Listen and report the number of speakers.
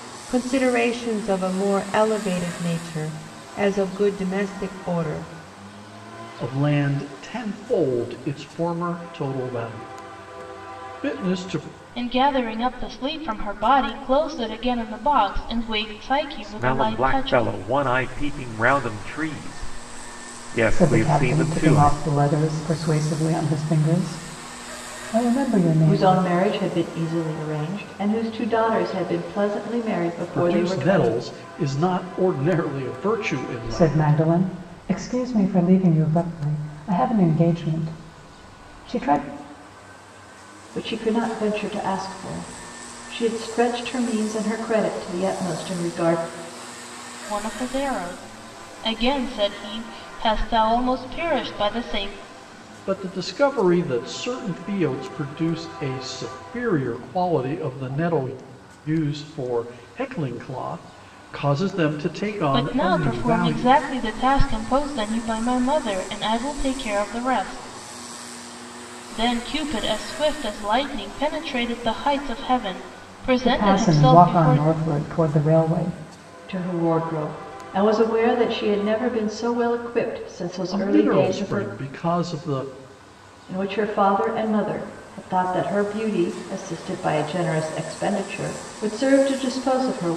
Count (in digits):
6